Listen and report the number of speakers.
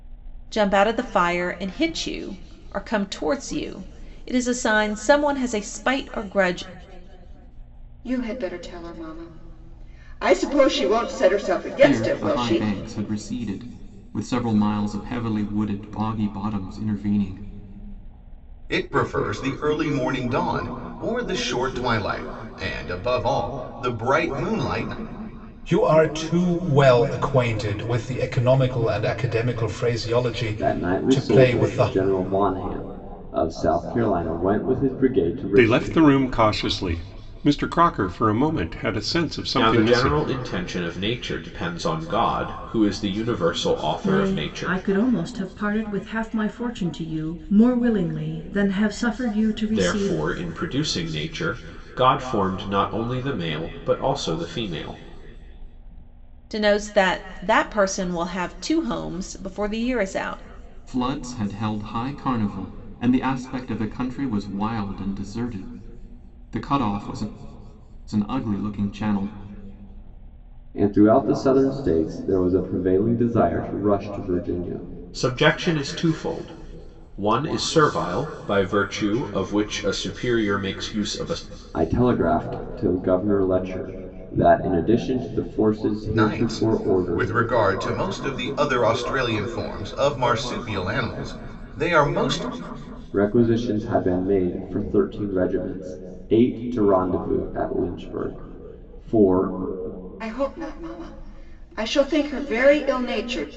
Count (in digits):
9